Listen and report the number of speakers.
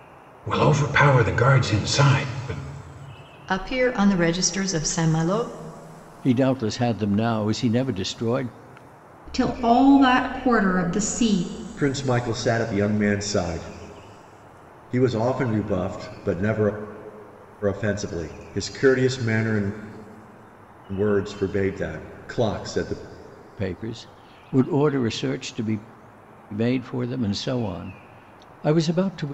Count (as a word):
five